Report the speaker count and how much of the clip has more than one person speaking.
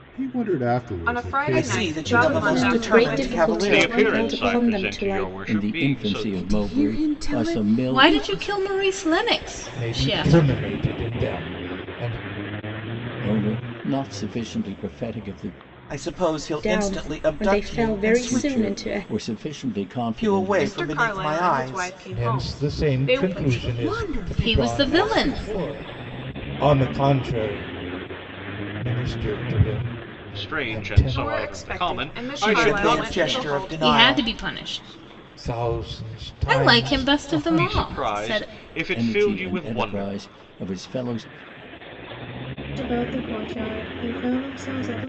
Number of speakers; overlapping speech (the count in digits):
10, about 52%